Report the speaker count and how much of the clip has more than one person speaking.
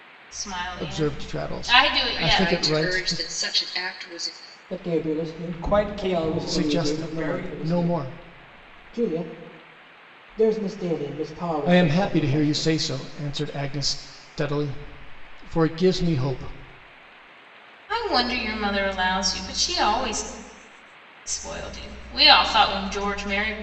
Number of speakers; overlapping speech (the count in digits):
5, about 27%